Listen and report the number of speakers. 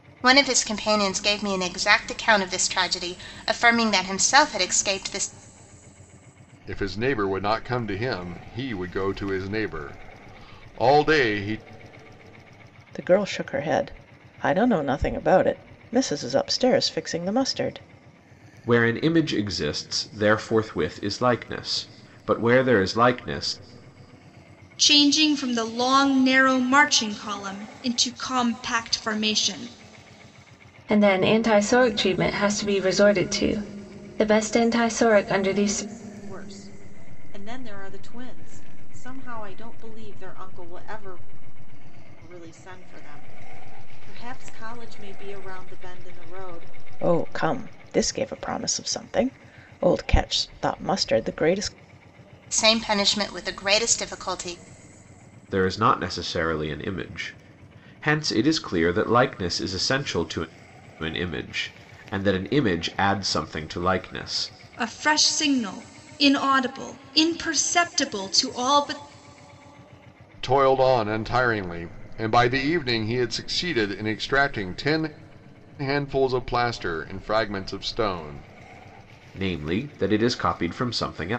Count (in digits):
7